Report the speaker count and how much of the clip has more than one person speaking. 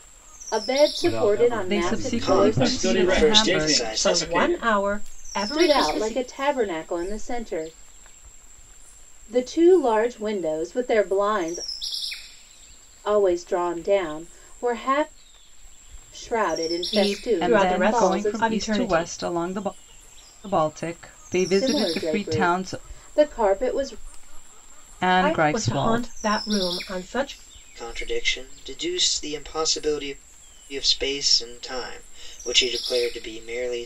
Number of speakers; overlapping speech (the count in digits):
6, about 26%